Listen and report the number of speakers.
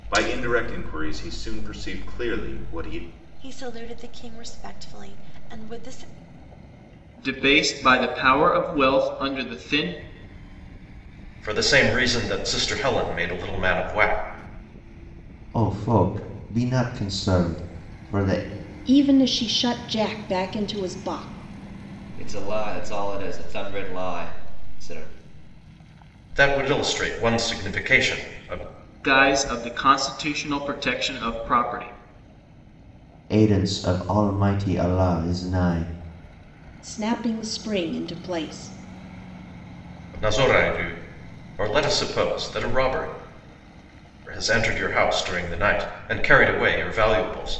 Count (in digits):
7